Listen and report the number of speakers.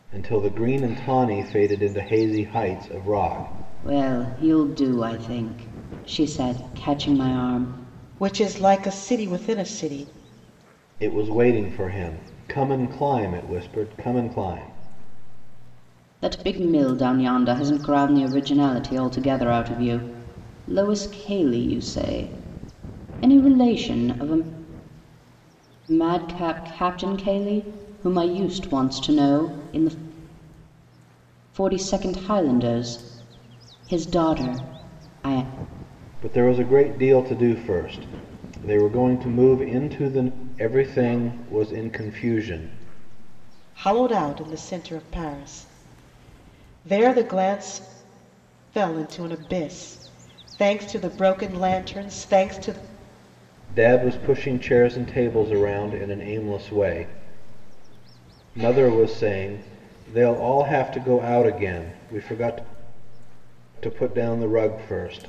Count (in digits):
3